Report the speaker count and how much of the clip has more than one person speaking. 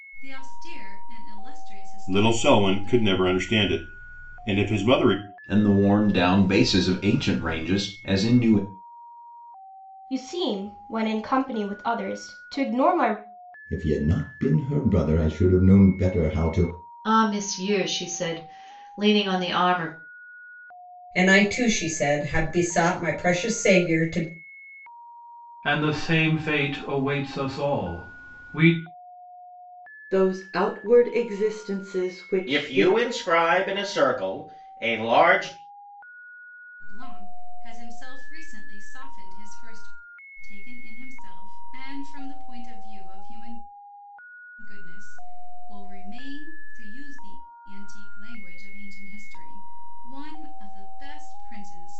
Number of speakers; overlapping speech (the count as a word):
ten, about 3%